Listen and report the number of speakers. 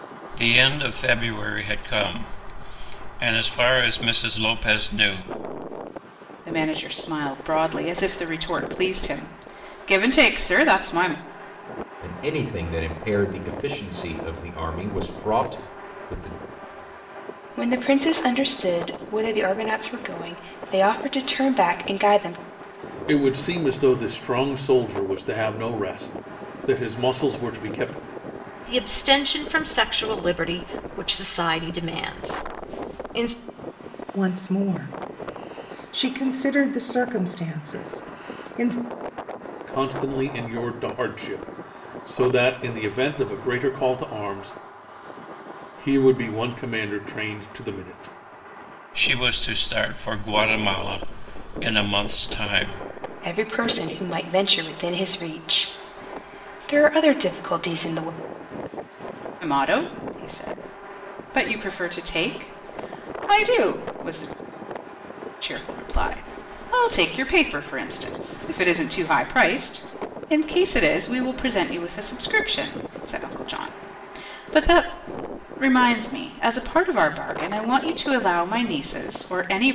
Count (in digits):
7